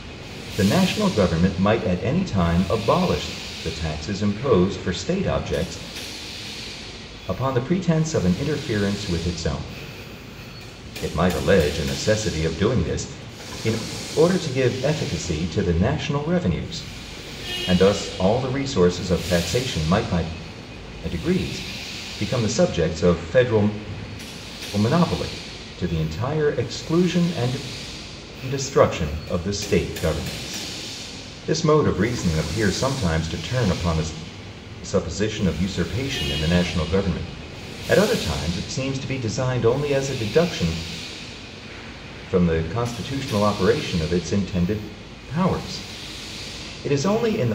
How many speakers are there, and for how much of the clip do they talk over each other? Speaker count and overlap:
1, no overlap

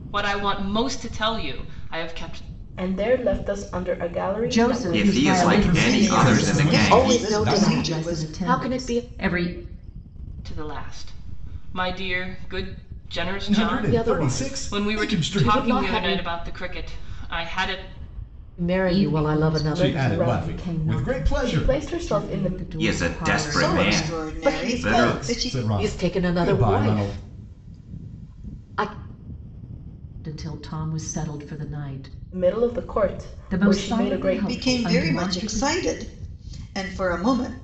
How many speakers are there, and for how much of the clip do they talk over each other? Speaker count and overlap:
7, about 47%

